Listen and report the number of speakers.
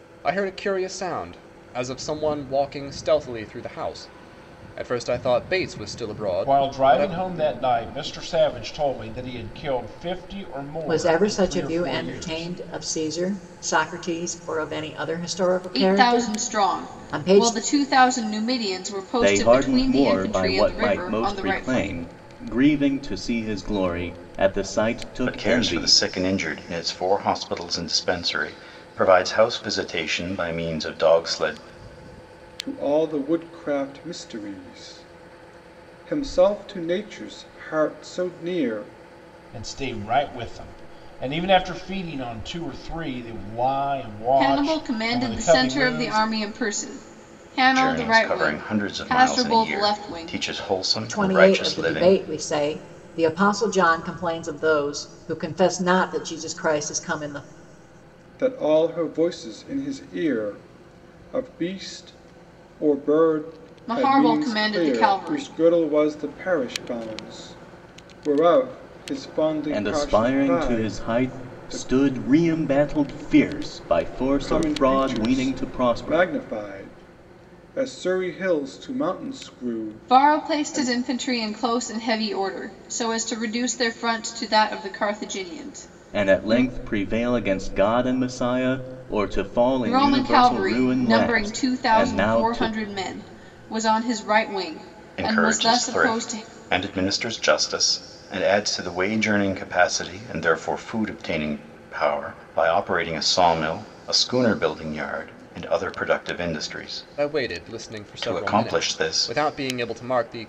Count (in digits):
7